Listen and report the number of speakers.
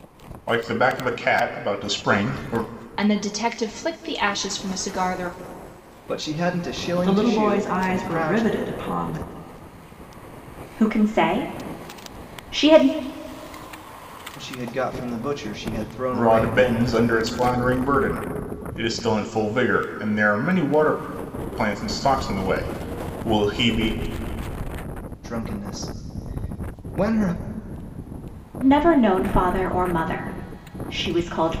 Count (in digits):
5